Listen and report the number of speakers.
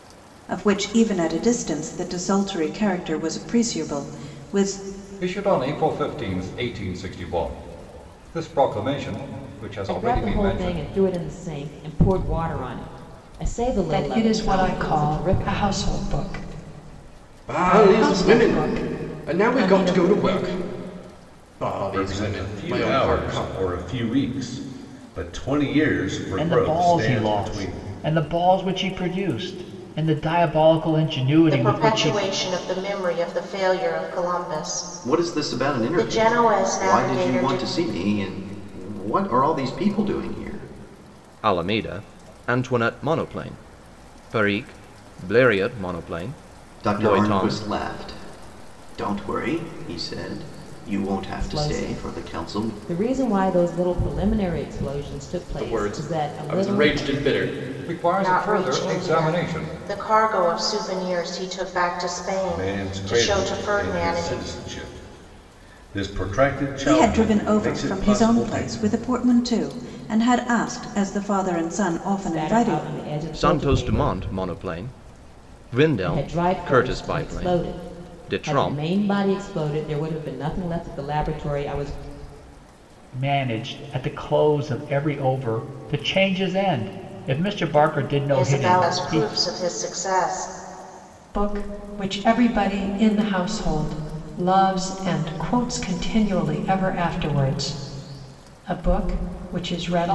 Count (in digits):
10